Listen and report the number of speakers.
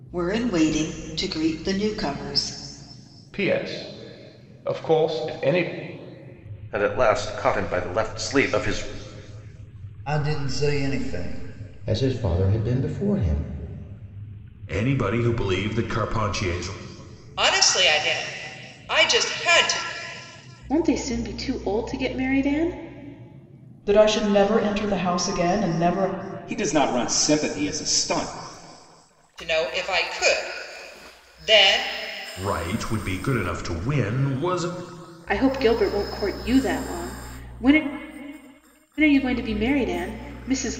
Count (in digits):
10